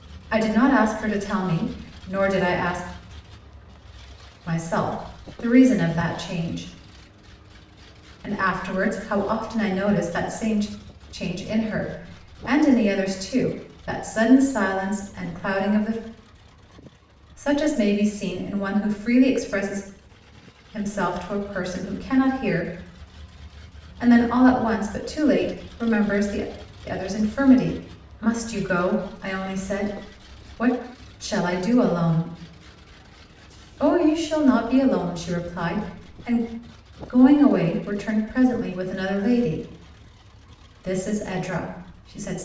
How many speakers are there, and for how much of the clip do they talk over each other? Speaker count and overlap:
1, no overlap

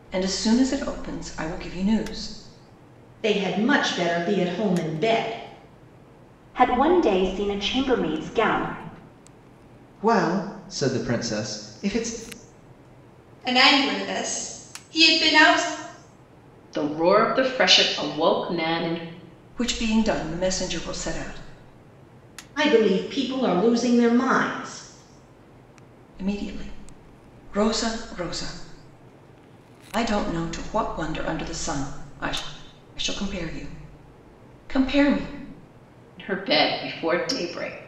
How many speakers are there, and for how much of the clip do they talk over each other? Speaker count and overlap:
6, no overlap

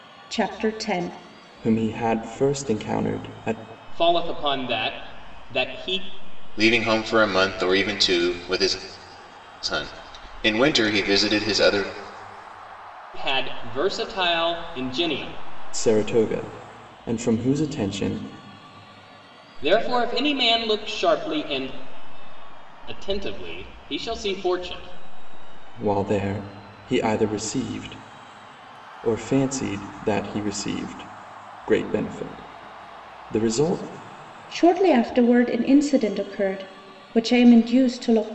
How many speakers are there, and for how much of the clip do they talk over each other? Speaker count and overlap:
4, no overlap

